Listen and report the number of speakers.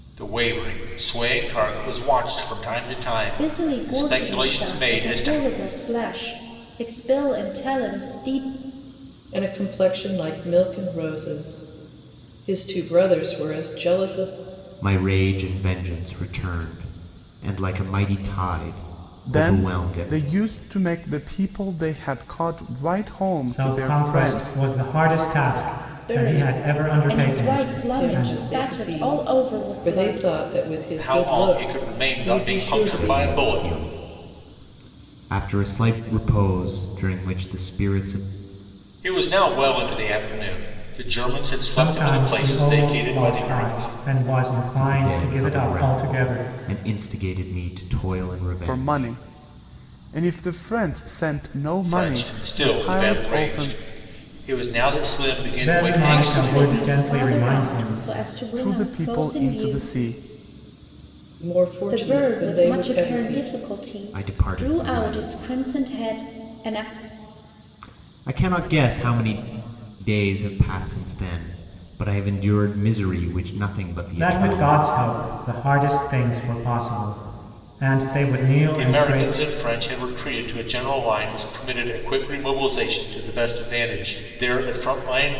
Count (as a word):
six